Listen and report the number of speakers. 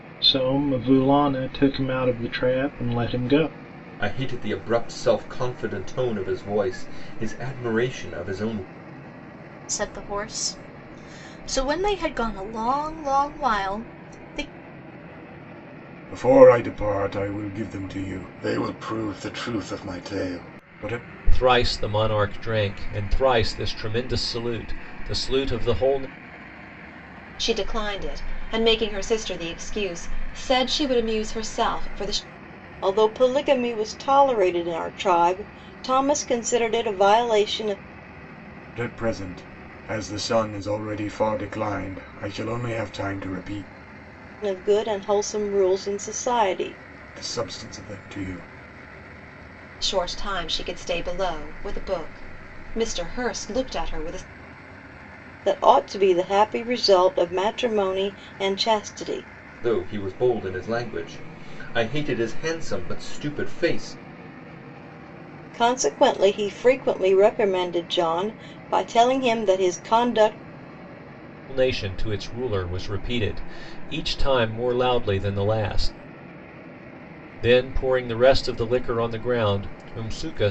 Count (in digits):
7